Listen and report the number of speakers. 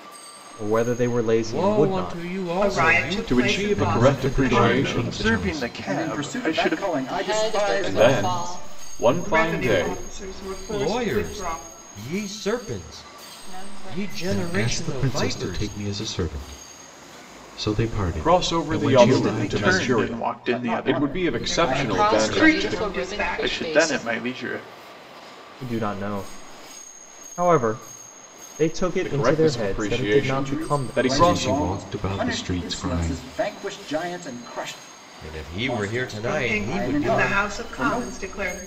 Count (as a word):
nine